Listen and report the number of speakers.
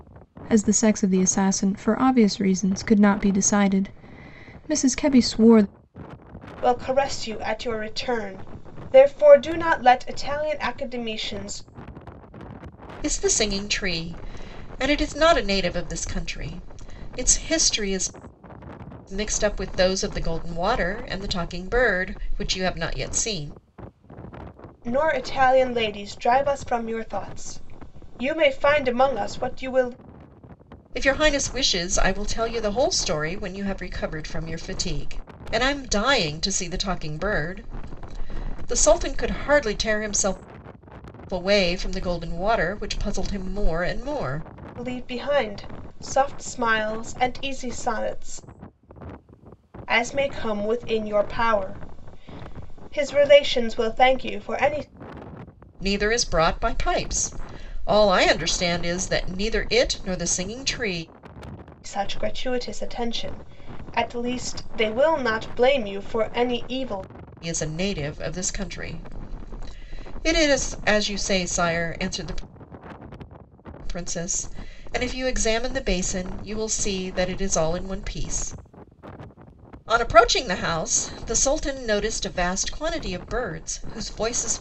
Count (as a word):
three